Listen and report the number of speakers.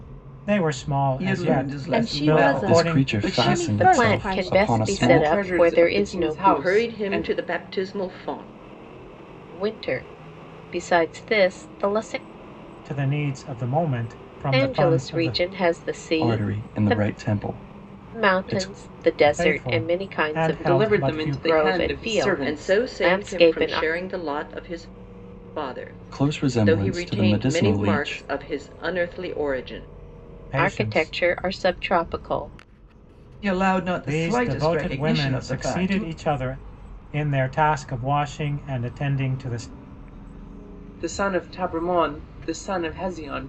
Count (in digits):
7